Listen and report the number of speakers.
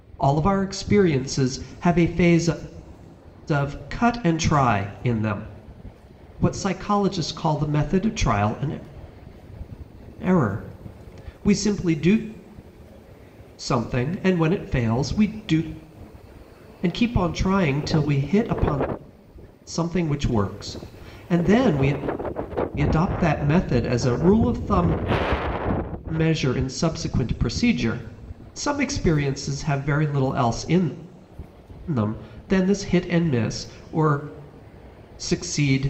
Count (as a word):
one